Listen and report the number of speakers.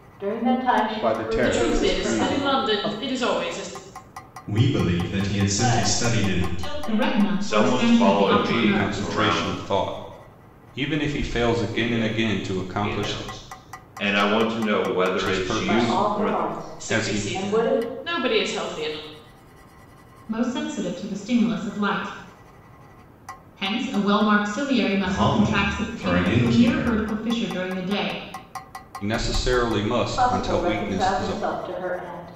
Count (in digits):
8